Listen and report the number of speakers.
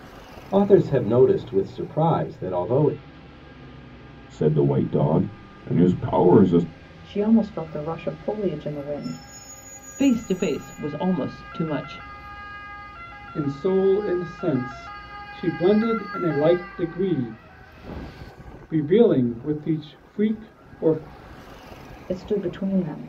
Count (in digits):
5